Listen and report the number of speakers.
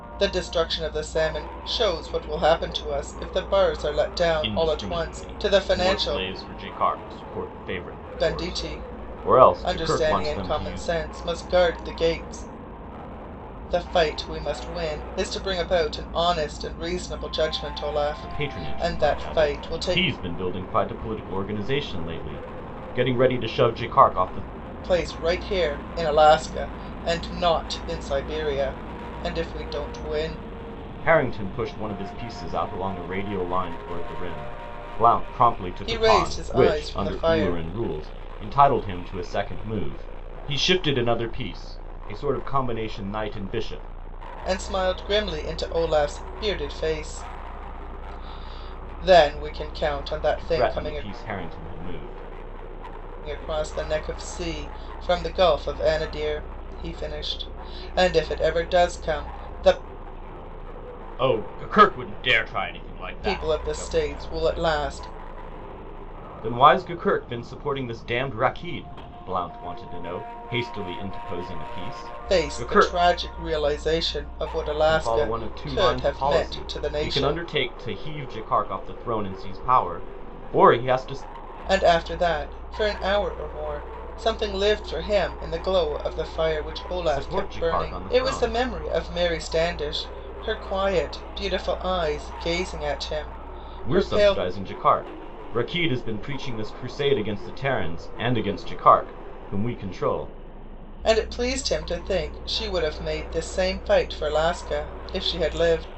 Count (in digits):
2